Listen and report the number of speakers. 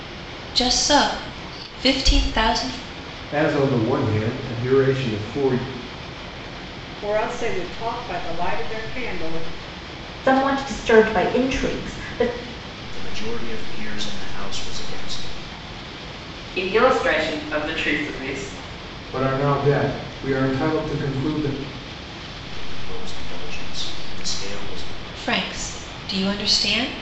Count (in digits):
7